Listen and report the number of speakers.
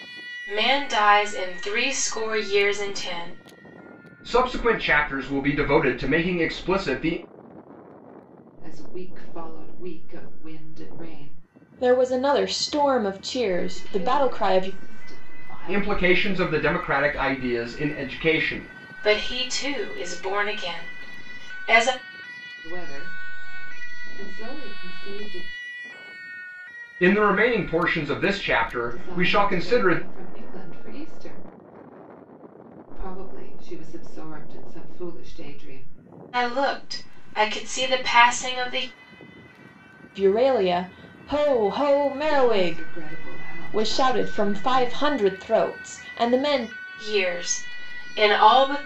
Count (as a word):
four